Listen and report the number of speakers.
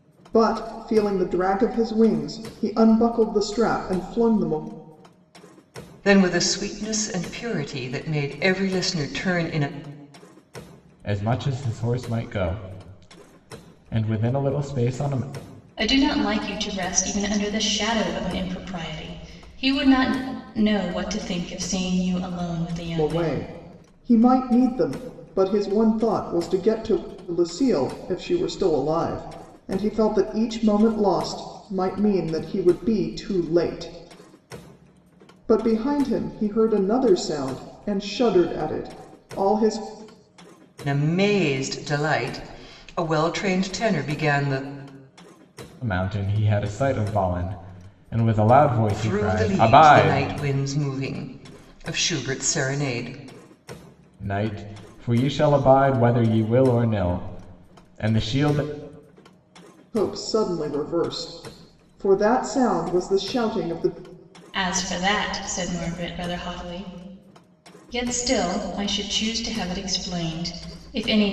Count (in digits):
4